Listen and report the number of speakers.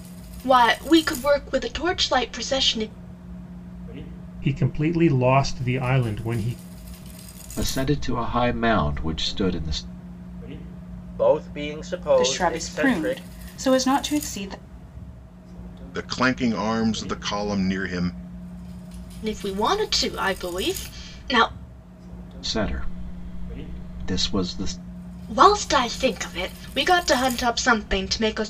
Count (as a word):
six